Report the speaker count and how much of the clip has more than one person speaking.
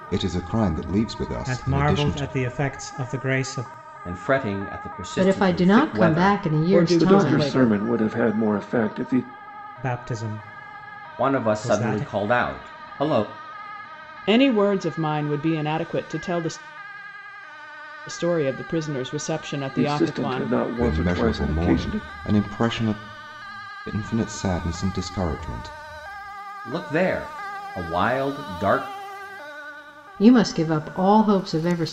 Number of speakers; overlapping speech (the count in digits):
6, about 19%